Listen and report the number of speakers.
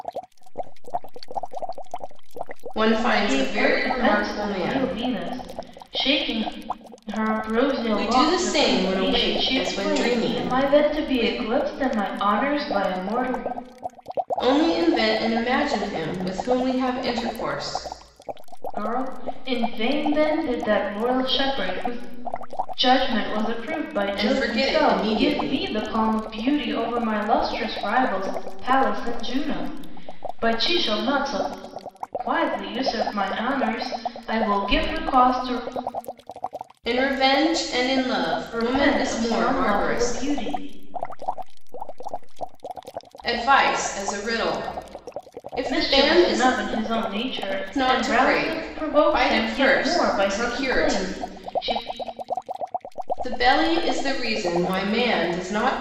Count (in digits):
3